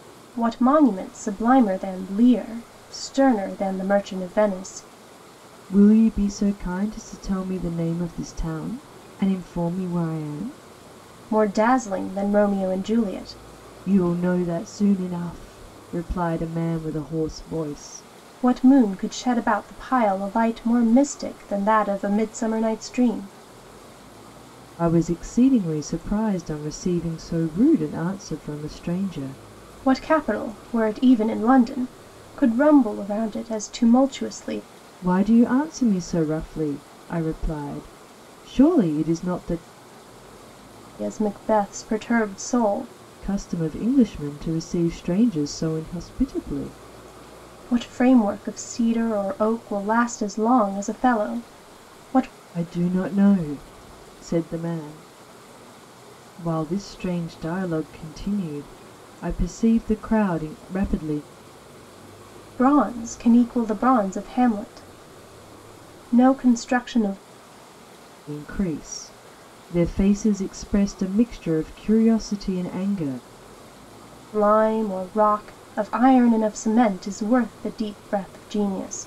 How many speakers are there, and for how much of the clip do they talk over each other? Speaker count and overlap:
2, no overlap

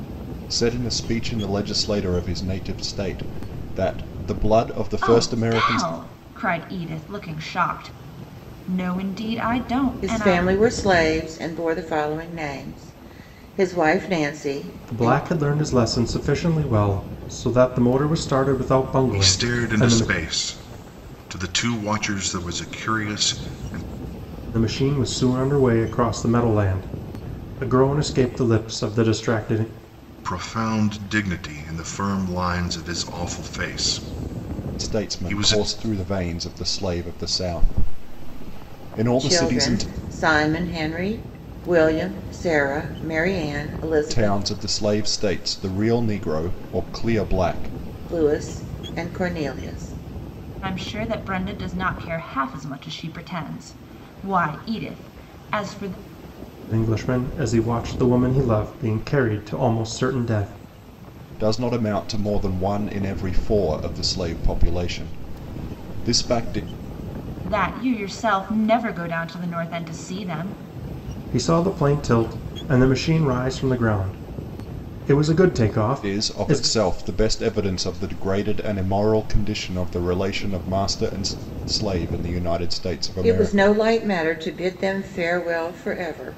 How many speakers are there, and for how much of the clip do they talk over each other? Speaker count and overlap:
5, about 7%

